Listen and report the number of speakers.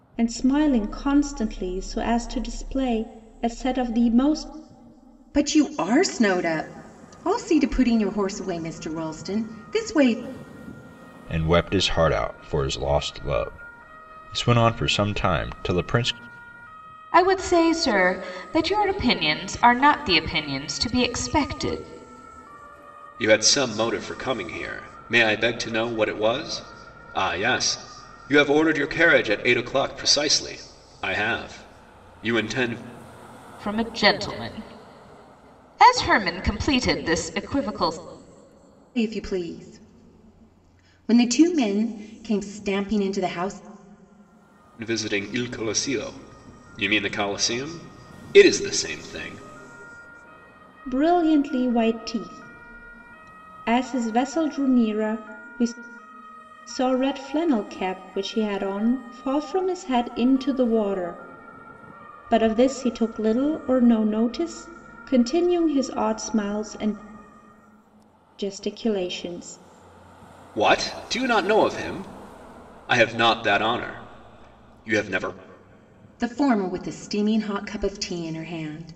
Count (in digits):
5